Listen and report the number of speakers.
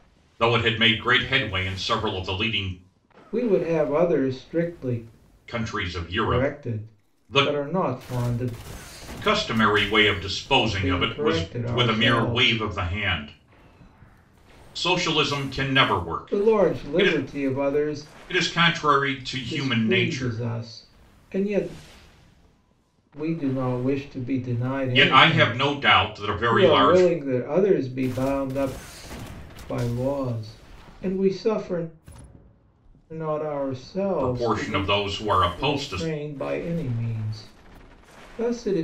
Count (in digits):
2